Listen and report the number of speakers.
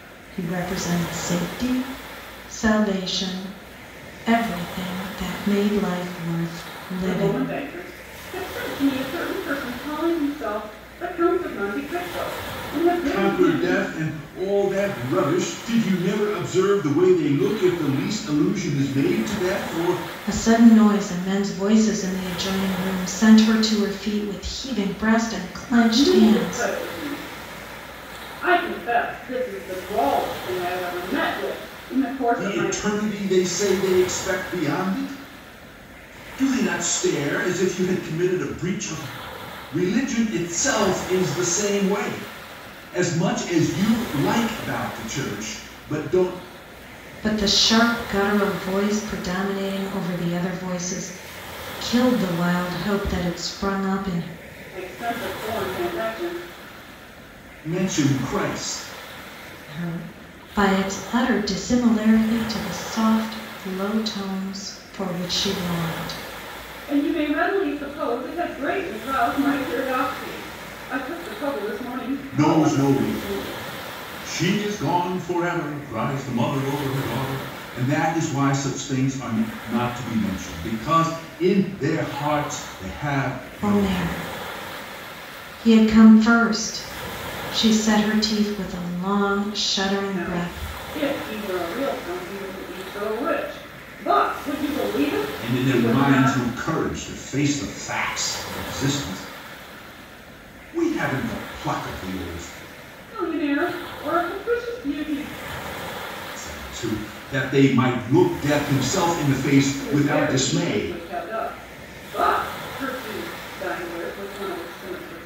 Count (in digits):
3